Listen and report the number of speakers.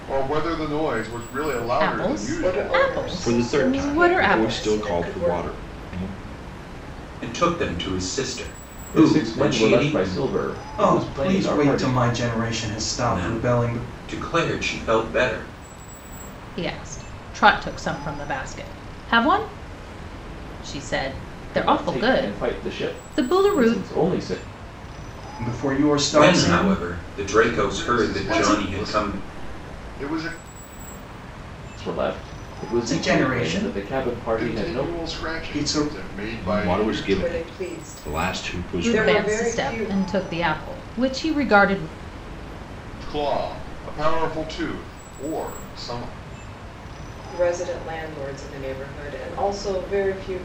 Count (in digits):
7